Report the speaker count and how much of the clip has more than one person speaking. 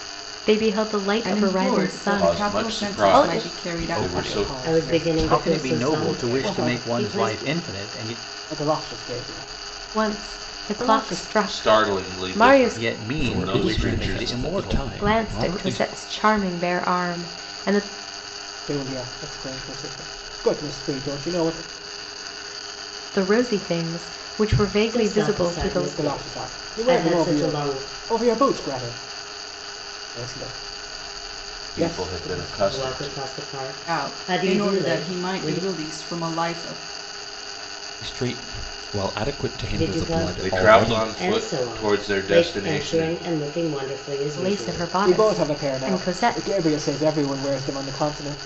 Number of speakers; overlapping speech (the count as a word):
seven, about 49%